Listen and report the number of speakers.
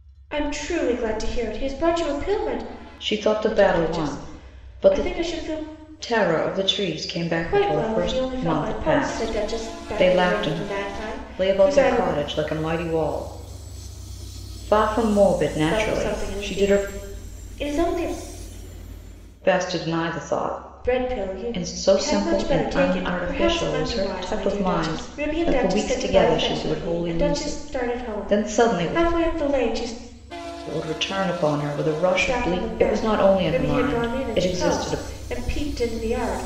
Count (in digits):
2